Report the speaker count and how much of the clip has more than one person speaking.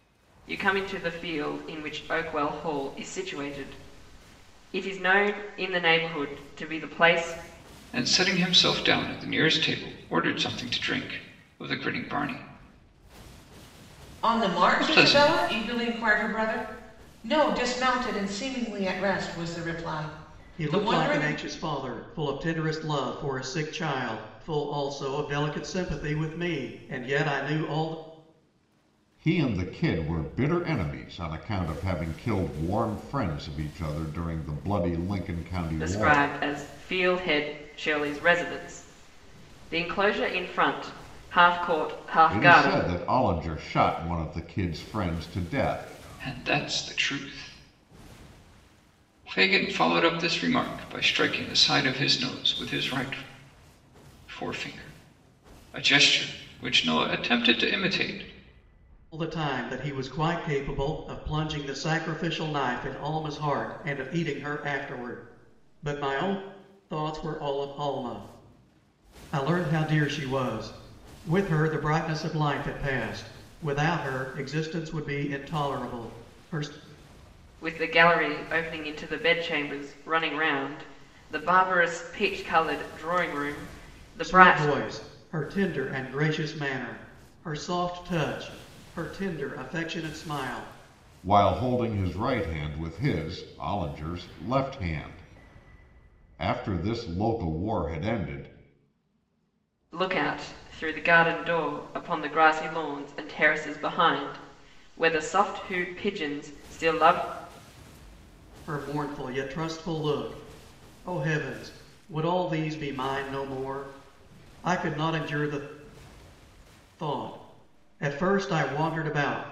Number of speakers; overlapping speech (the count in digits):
5, about 3%